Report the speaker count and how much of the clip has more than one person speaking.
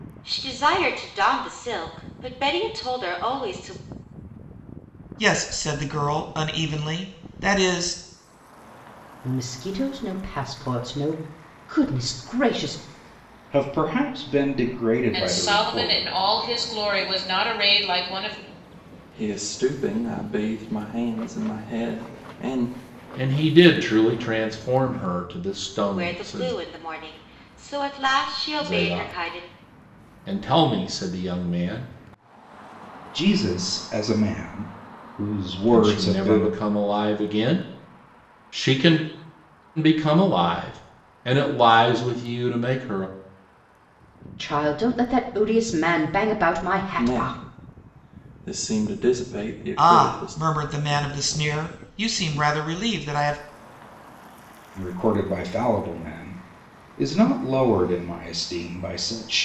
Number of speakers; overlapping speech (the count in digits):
7, about 8%